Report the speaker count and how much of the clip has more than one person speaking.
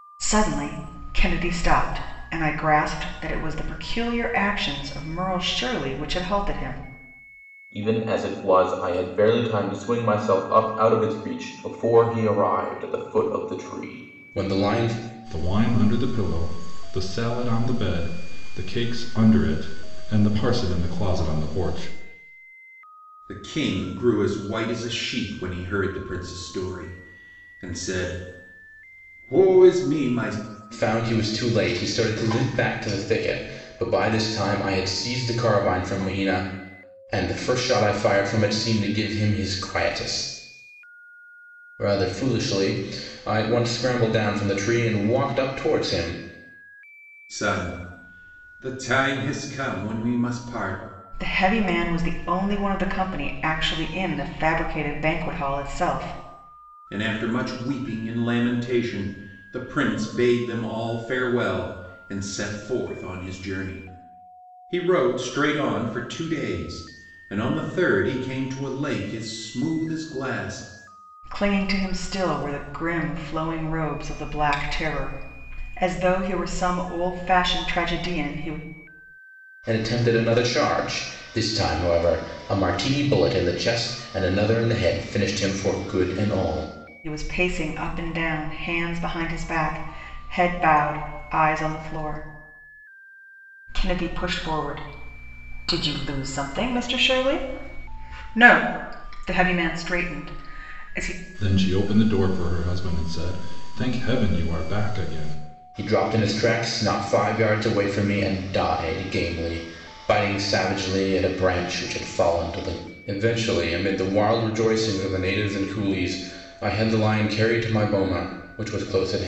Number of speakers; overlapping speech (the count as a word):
four, no overlap